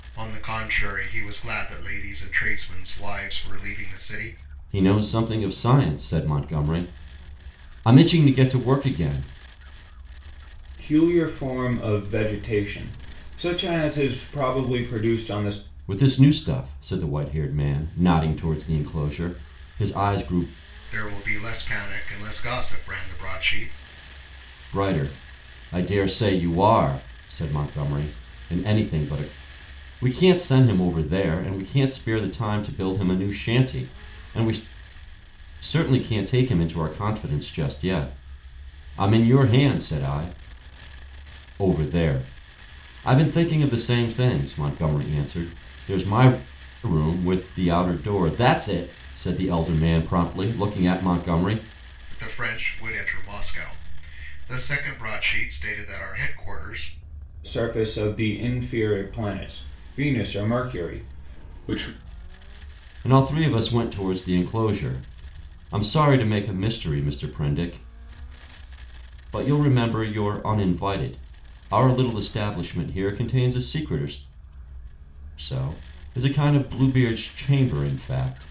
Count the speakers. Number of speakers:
3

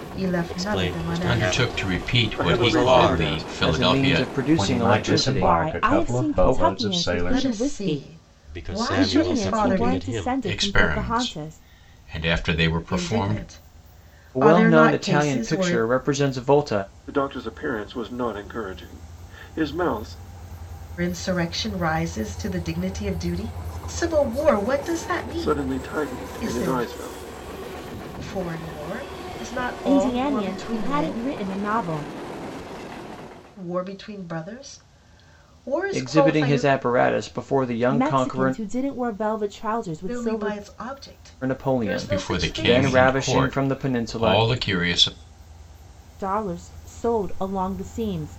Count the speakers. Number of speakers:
7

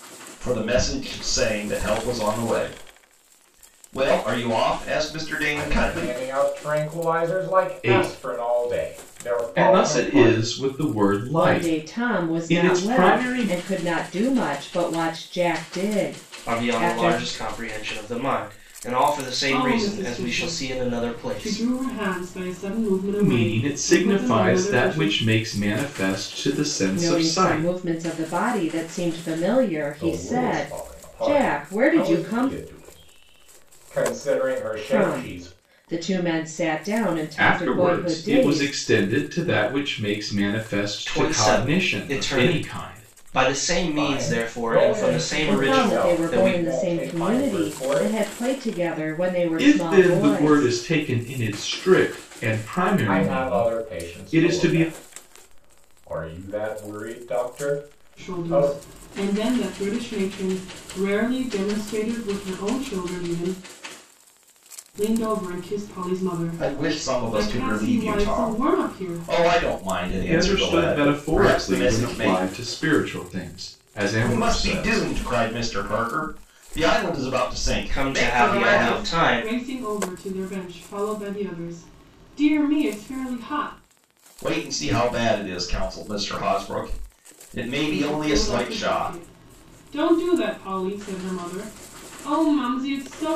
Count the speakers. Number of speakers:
6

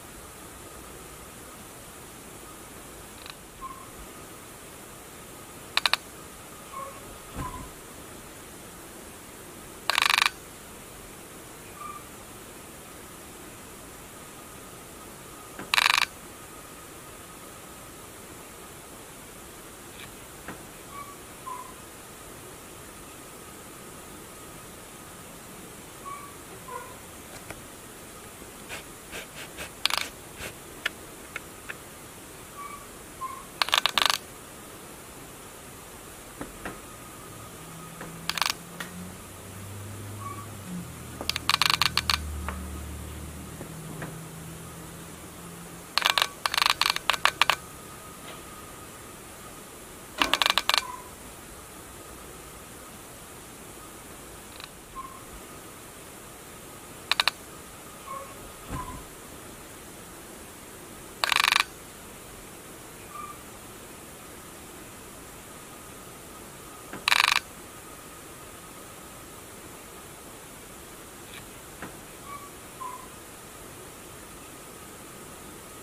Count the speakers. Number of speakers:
0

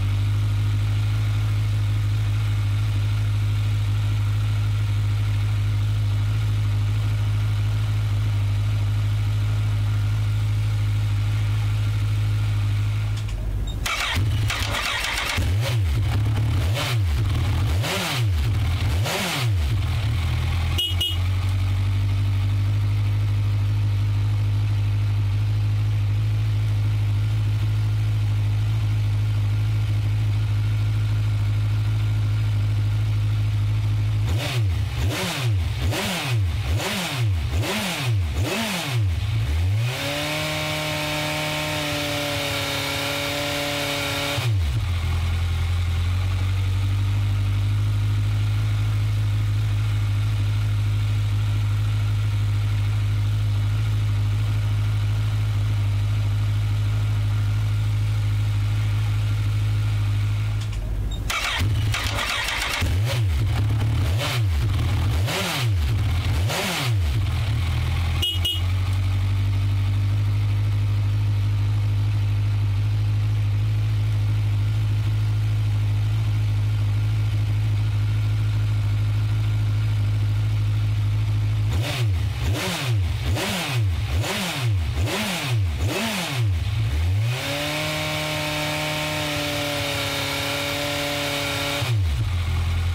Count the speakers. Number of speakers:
0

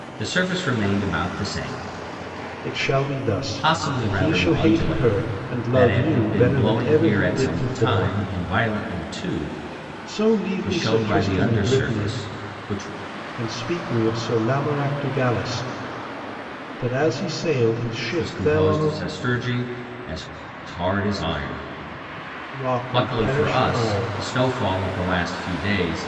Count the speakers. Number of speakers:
2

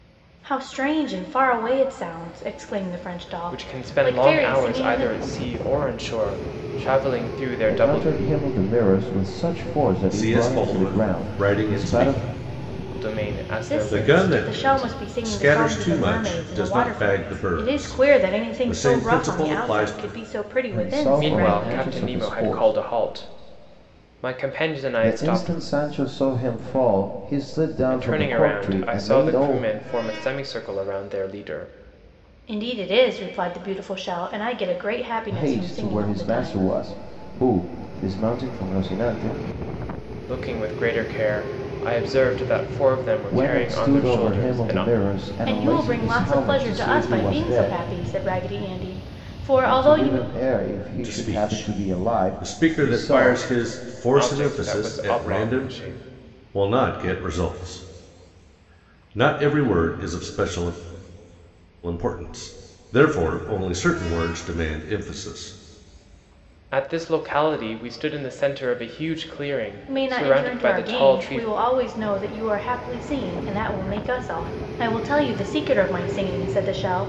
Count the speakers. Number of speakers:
4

